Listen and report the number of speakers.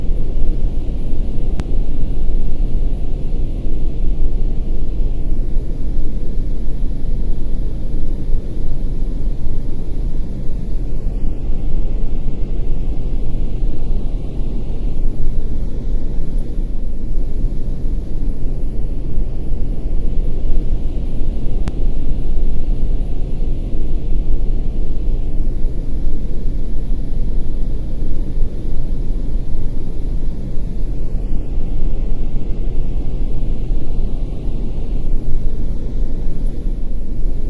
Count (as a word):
zero